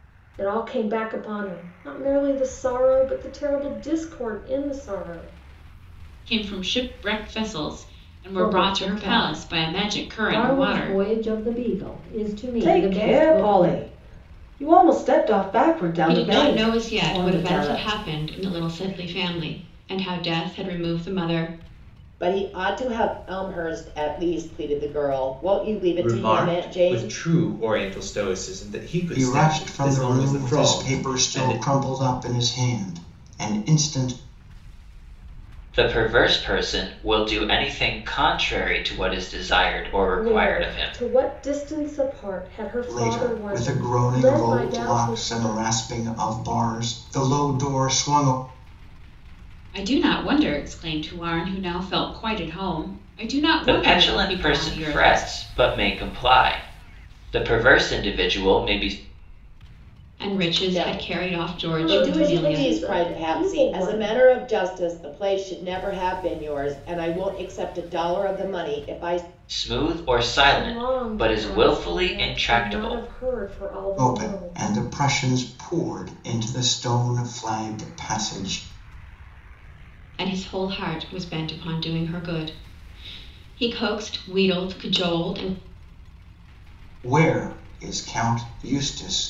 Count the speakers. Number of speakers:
nine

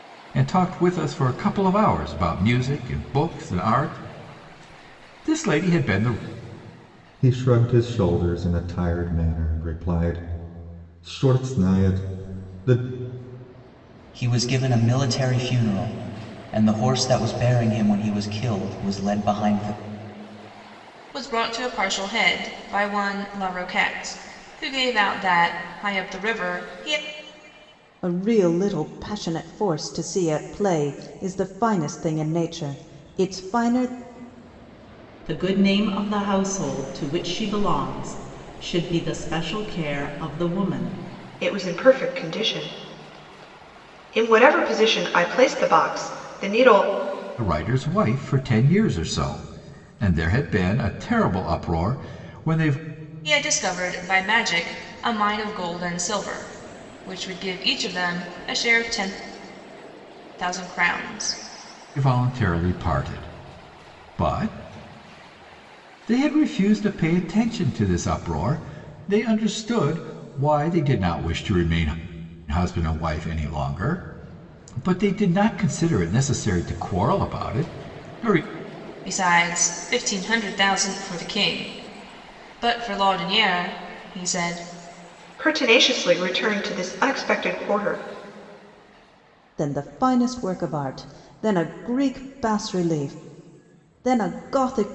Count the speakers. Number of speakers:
seven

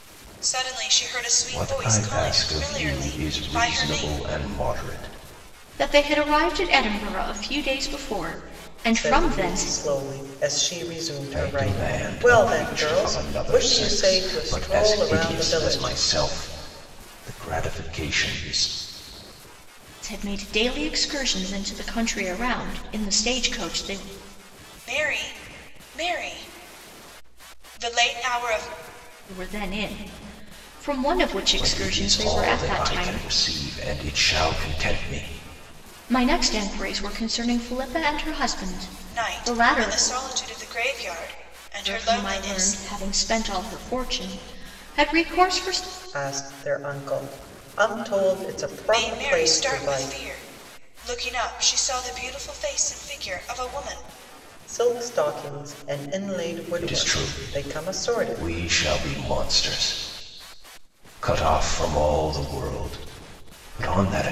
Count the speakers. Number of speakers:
four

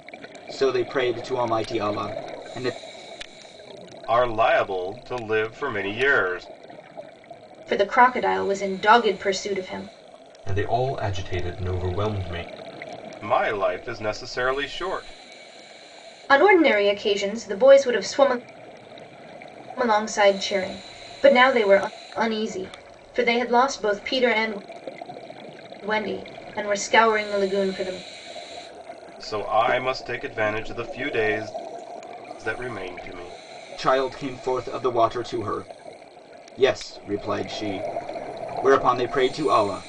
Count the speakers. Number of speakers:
four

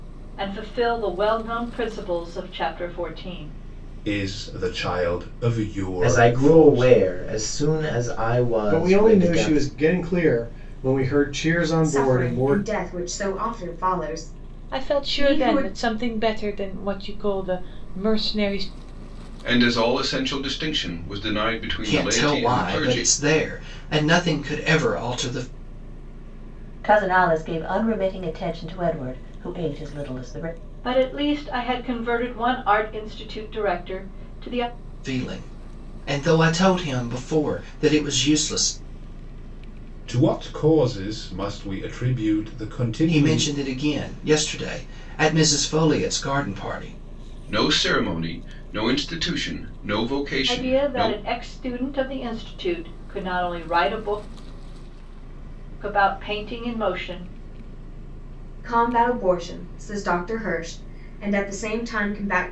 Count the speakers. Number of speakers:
nine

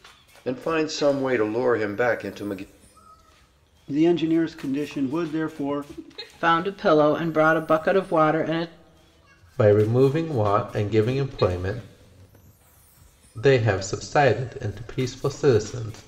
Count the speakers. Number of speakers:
four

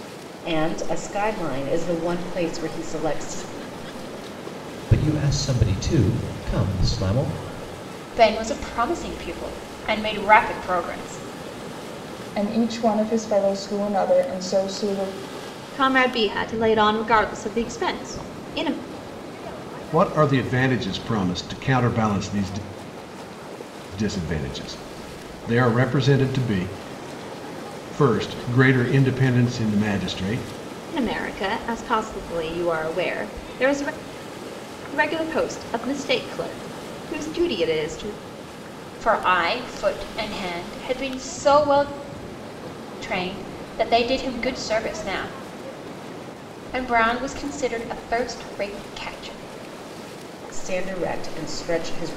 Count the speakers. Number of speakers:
six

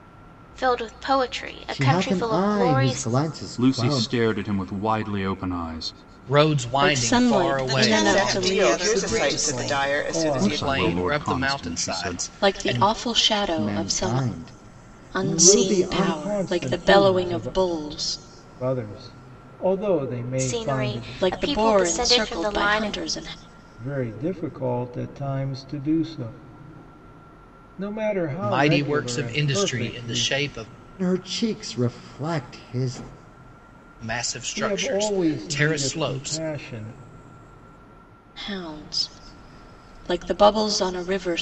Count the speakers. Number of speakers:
eight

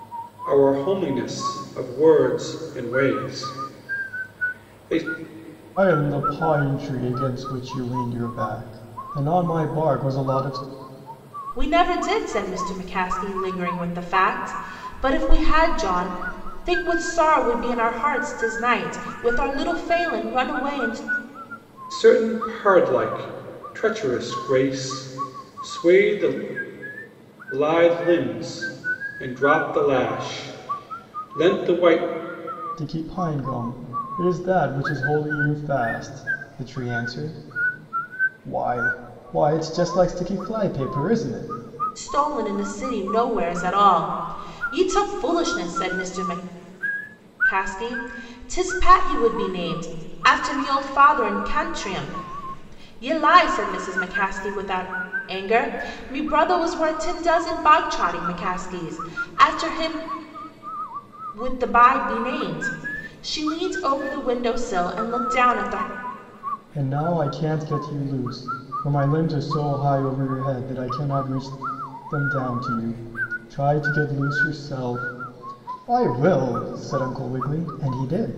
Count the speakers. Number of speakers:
three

